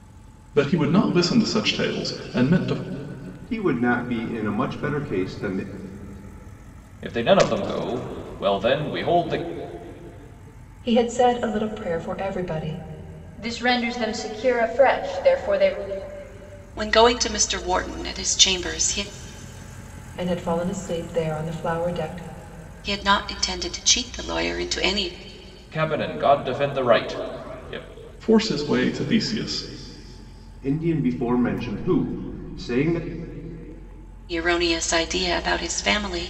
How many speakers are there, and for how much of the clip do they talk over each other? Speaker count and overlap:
6, no overlap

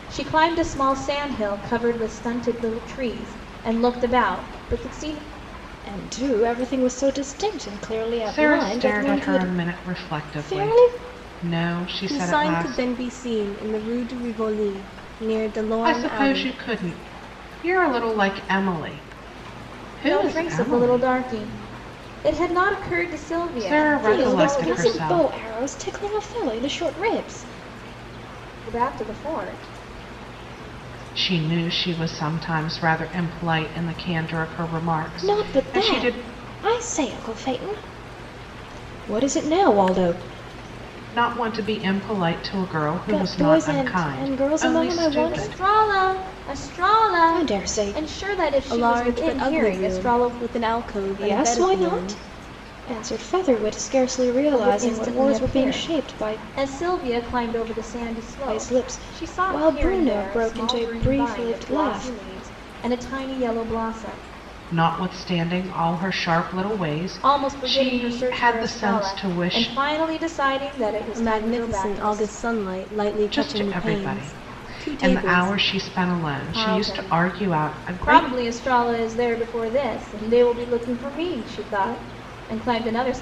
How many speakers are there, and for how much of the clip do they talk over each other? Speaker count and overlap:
4, about 35%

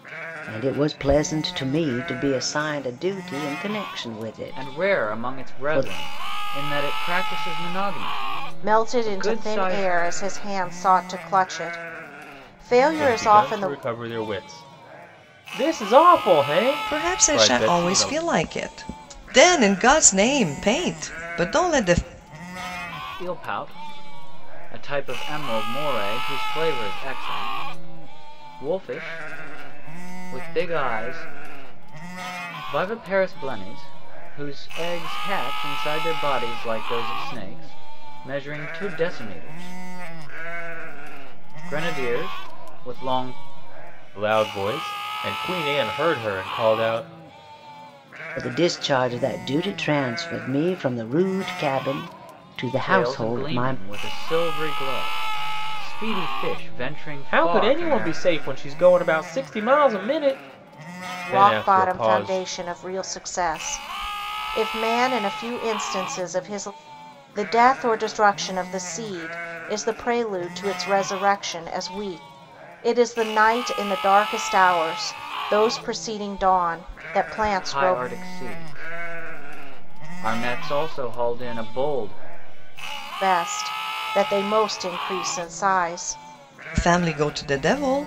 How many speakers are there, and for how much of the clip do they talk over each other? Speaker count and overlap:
5, about 10%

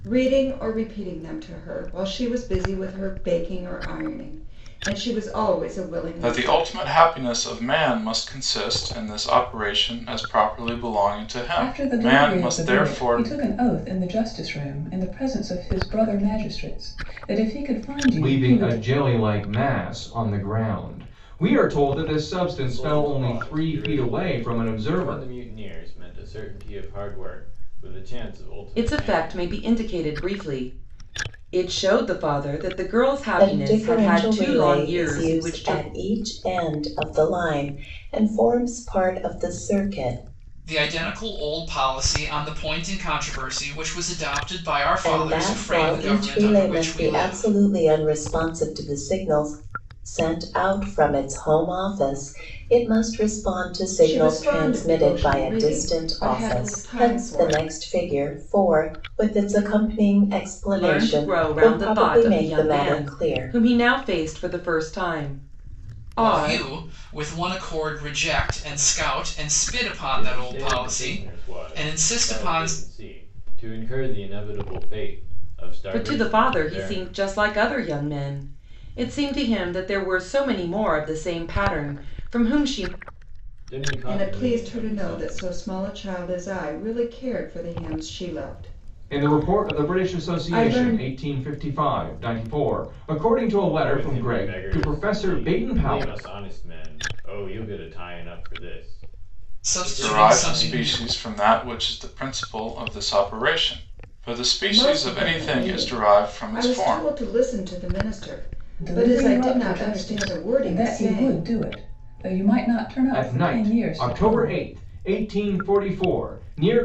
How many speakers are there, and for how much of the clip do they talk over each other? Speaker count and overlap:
8, about 31%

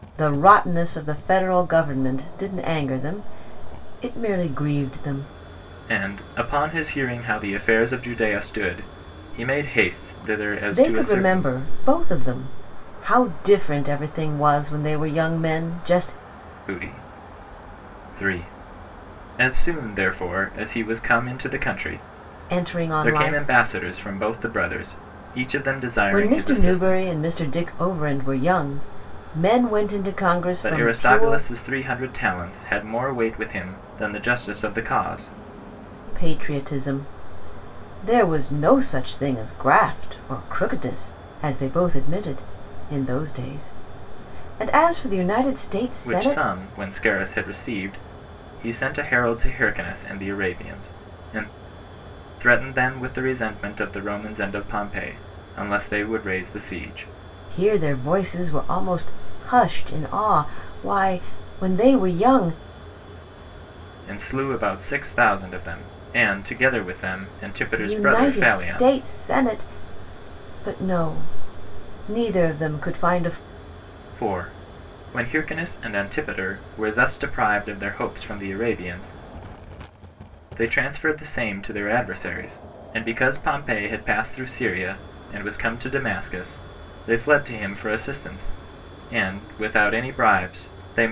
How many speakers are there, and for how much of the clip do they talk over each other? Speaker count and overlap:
2, about 6%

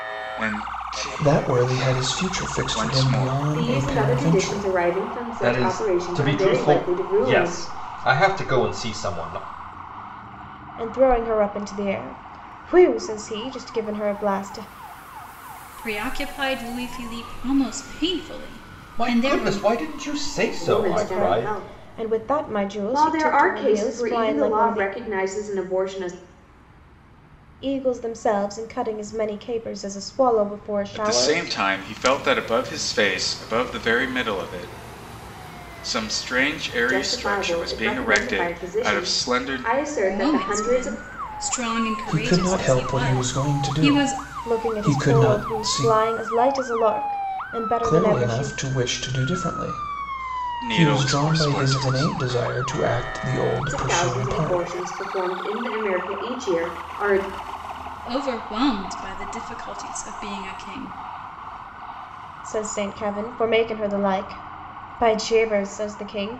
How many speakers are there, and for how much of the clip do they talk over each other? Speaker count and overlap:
6, about 32%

